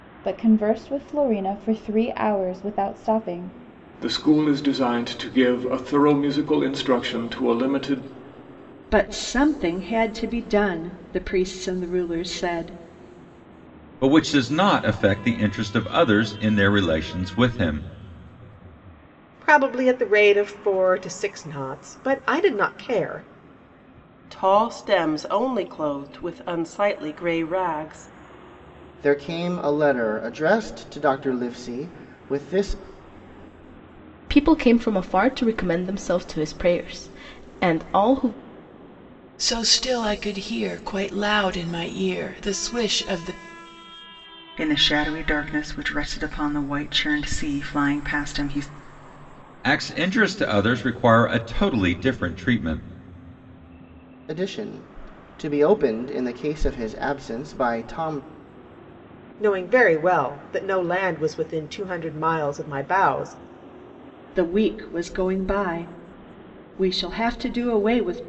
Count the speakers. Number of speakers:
ten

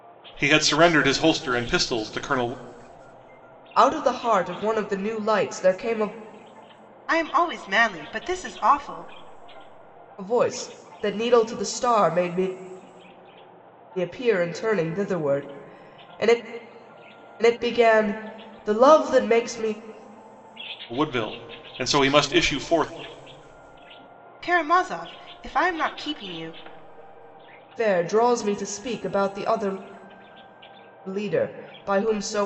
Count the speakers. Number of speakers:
three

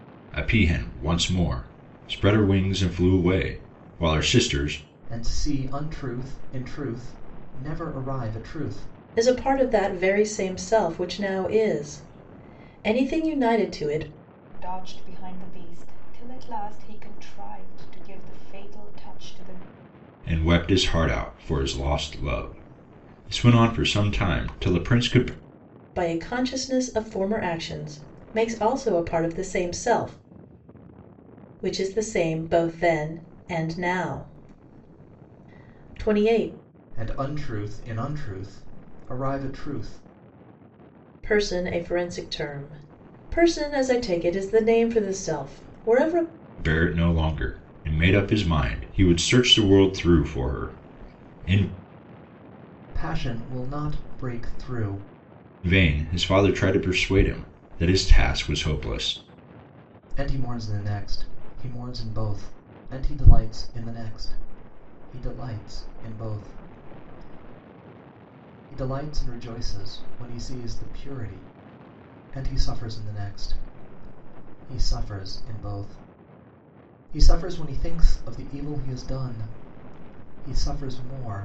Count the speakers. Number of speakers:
four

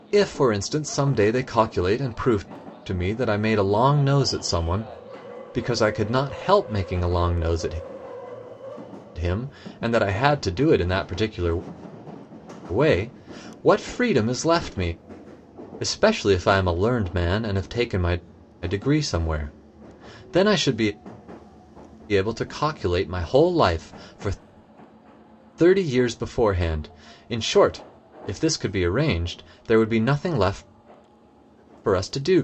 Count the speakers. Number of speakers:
one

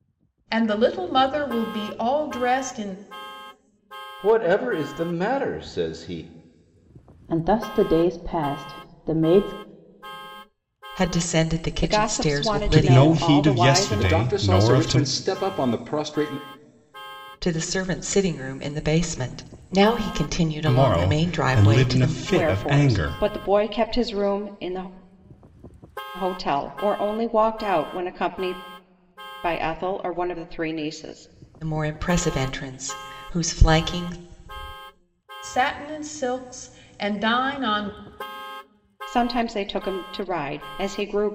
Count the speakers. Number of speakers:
seven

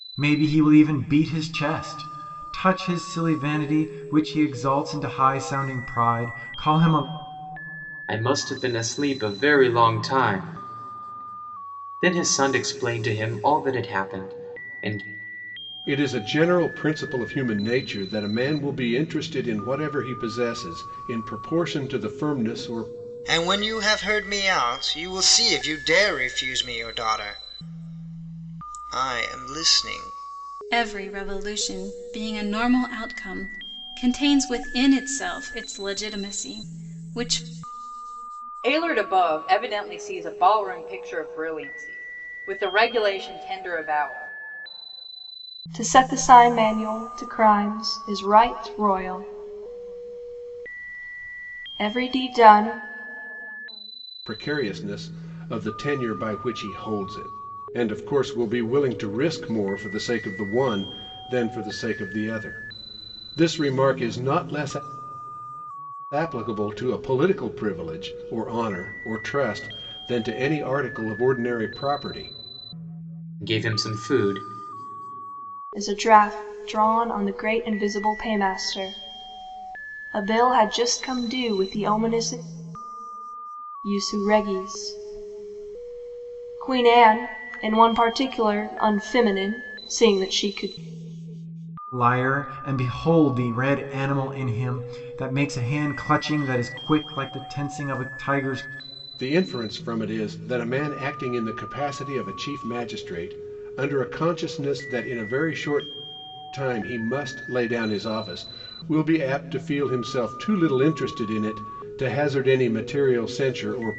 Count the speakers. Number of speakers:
seven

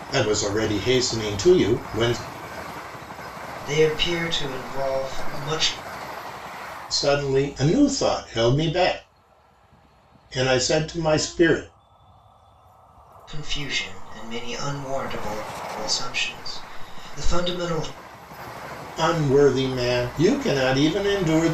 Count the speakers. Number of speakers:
two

